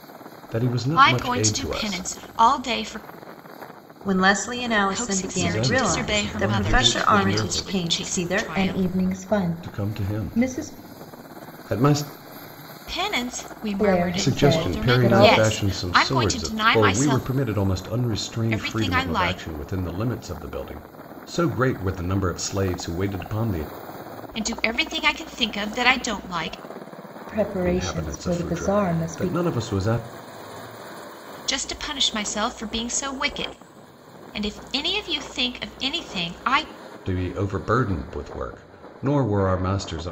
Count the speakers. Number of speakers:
3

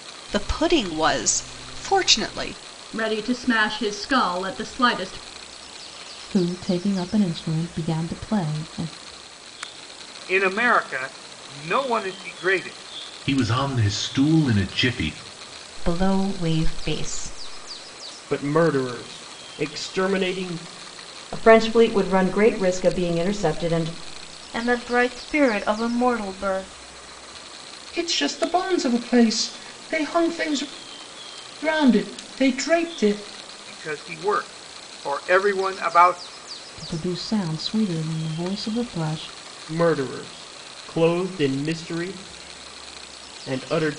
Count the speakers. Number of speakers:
10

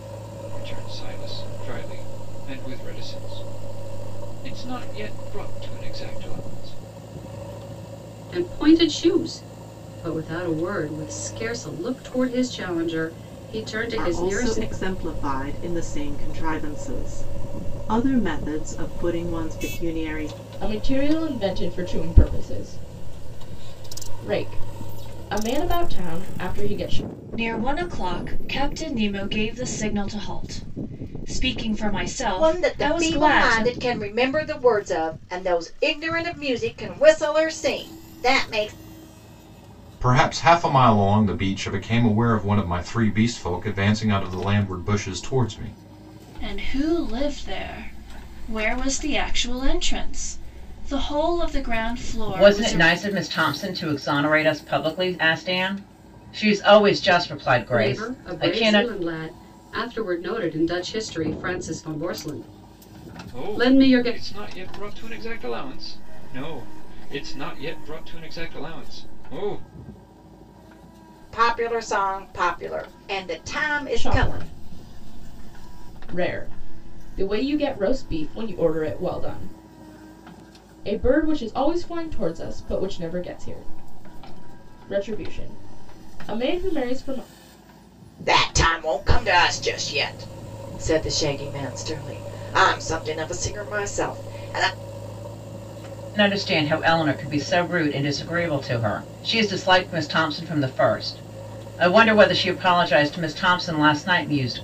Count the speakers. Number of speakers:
9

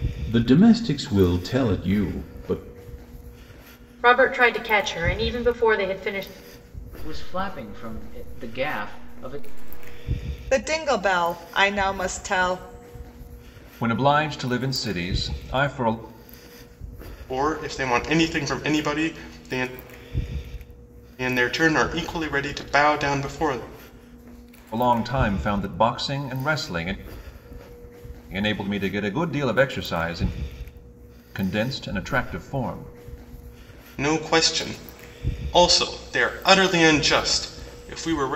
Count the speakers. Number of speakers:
6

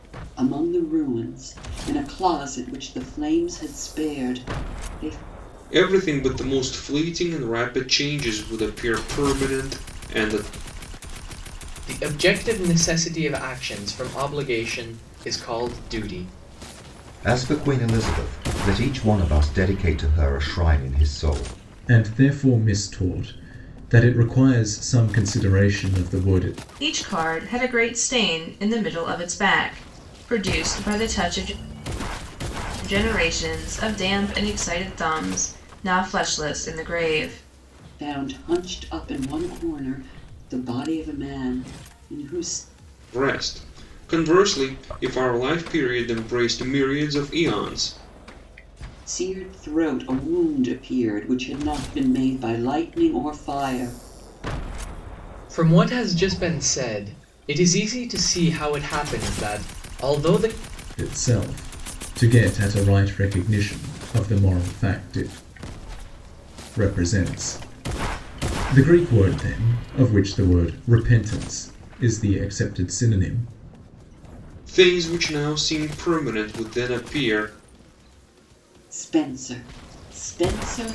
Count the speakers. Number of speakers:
6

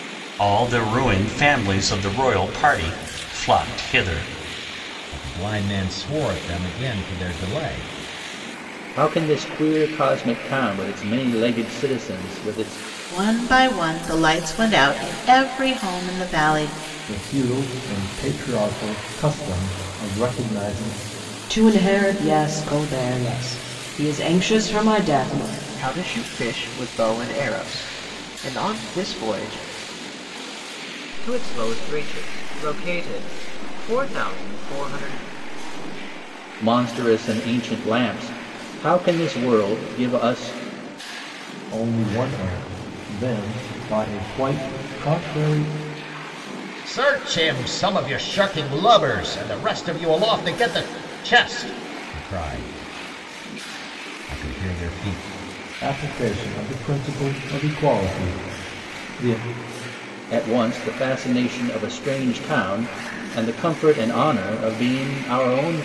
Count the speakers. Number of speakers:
8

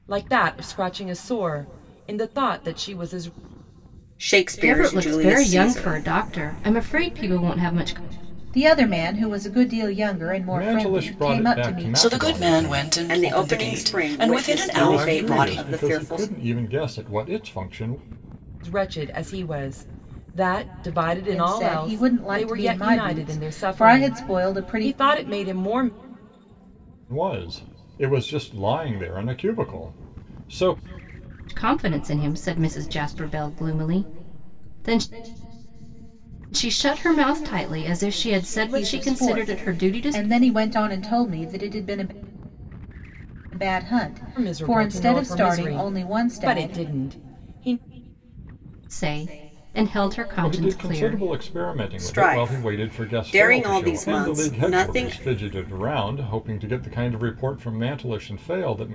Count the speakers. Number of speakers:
6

